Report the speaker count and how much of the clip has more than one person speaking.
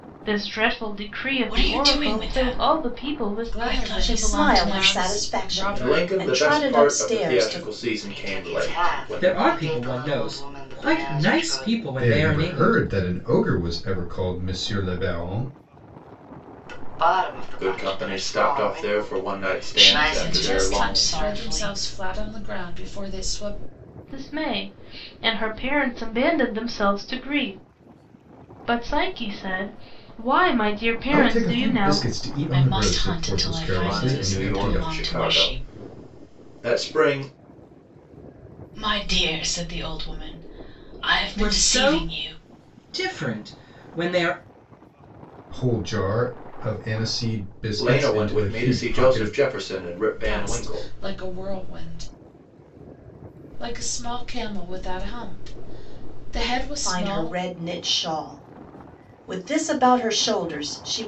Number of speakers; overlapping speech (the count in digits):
8, about 38%